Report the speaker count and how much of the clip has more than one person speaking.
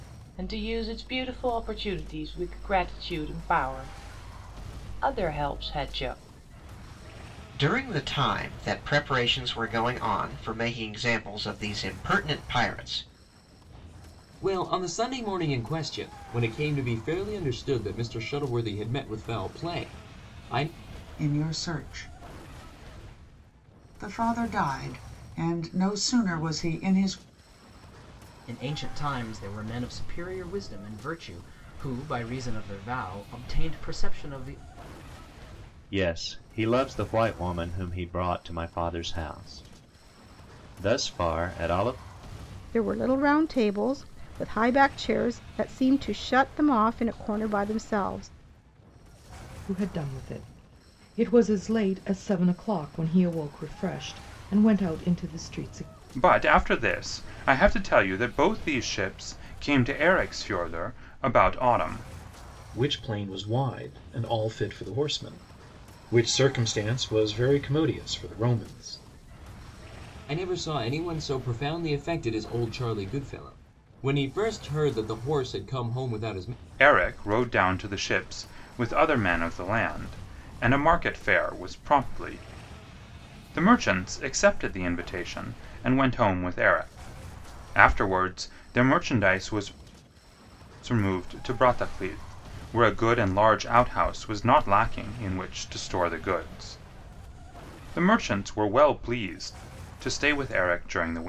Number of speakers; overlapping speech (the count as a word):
ten, no overlap